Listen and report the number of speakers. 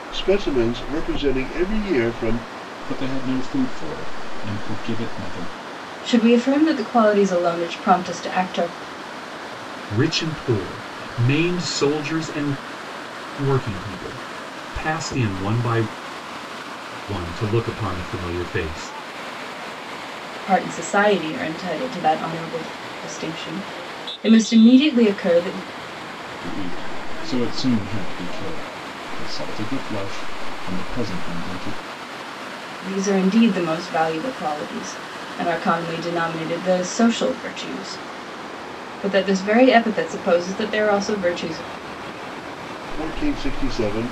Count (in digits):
4